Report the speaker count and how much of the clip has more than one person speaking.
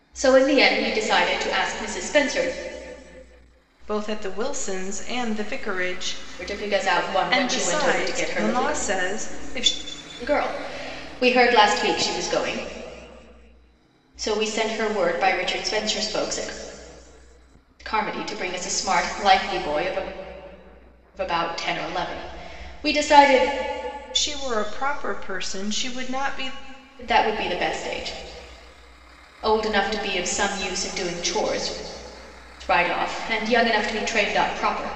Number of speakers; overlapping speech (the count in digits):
2, about 4%